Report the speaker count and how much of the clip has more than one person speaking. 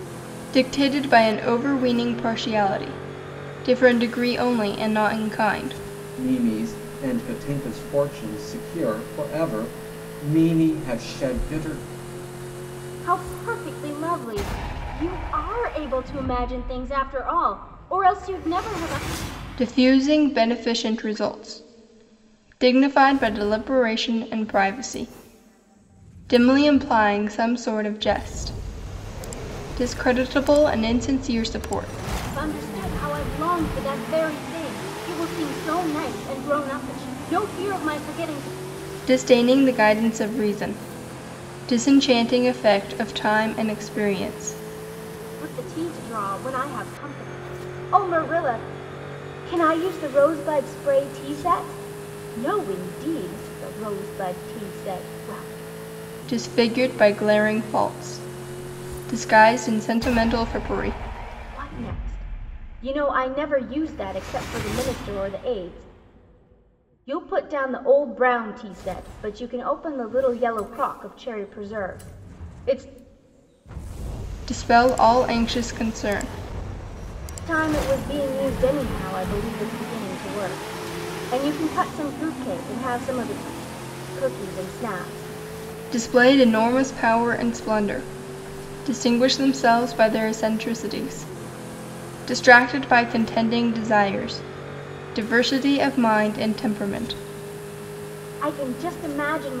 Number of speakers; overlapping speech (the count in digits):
3, no overlap